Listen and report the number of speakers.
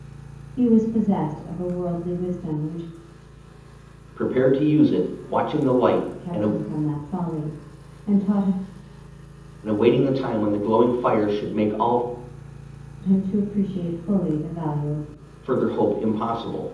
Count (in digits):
2